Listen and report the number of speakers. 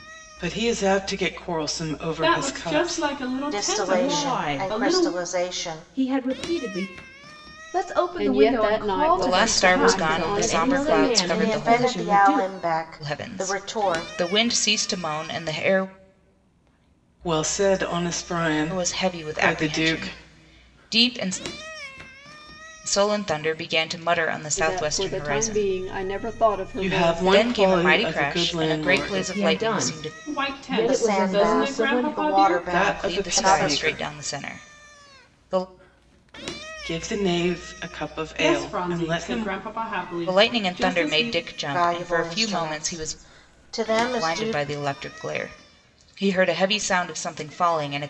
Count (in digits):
7